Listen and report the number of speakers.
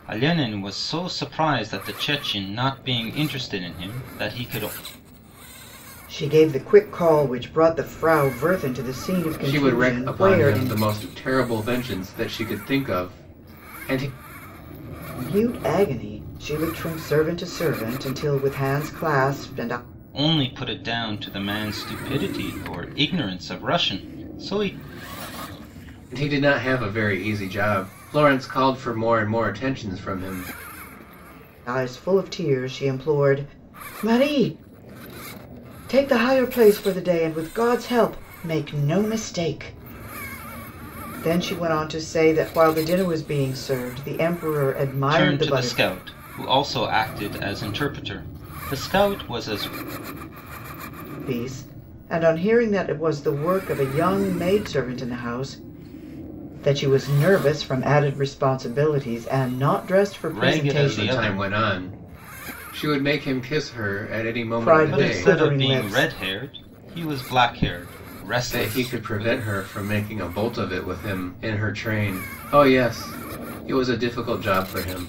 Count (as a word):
three